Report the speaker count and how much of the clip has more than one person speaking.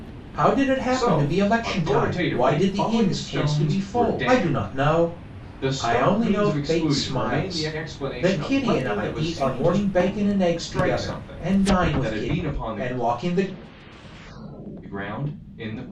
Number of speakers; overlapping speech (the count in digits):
2, about 64%